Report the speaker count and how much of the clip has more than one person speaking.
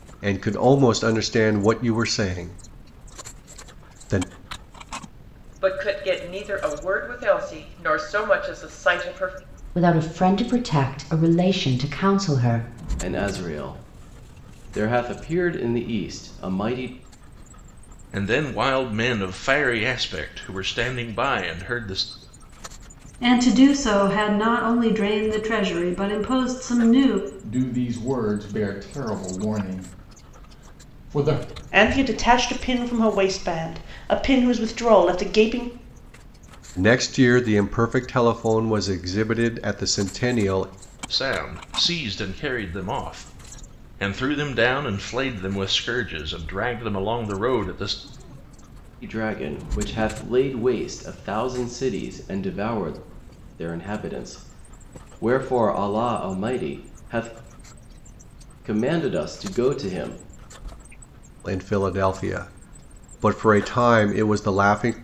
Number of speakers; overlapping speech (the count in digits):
8, no overlap